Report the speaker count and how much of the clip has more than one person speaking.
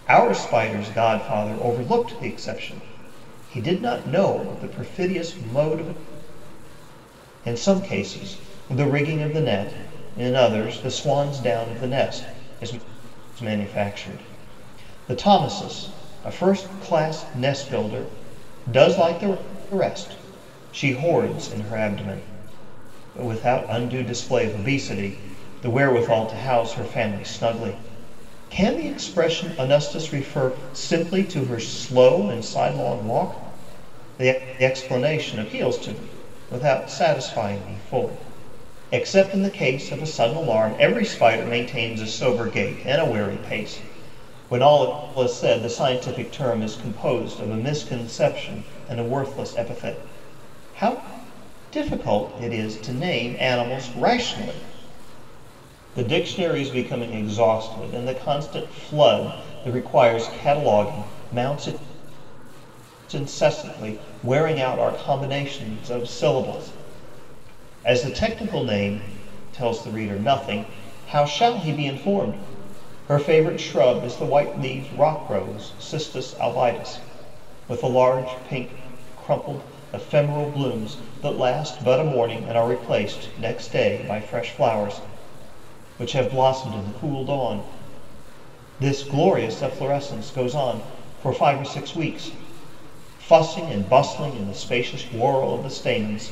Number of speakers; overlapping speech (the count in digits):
1, no overlap